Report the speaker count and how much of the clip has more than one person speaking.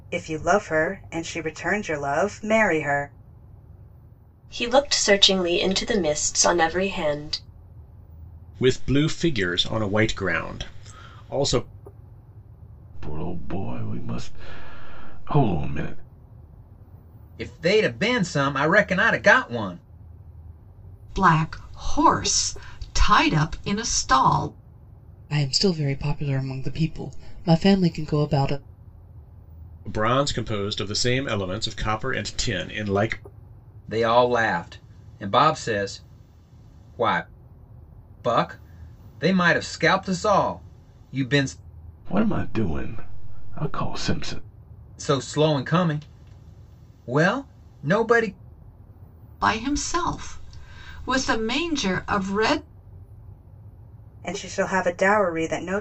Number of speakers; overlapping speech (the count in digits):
7, no overlap